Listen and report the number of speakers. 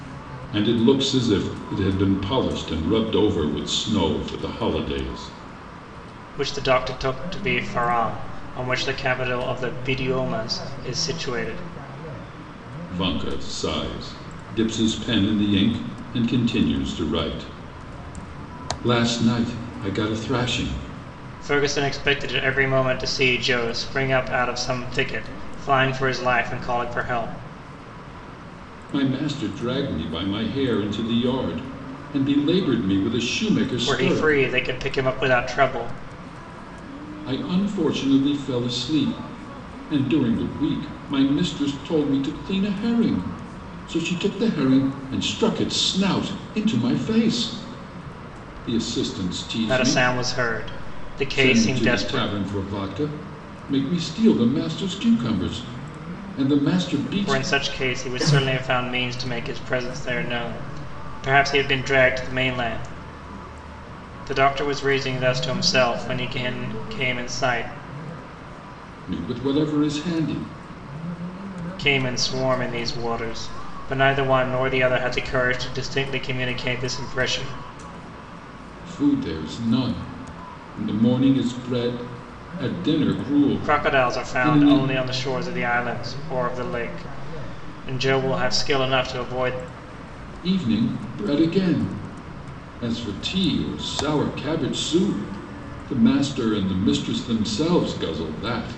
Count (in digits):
2